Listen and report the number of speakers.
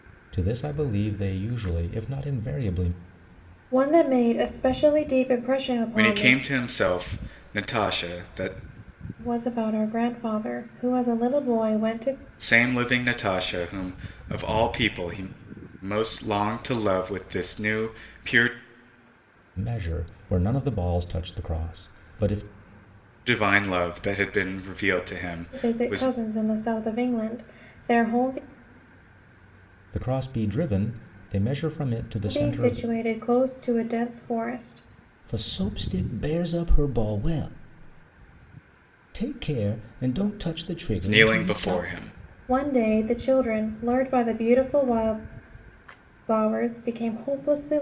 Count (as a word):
three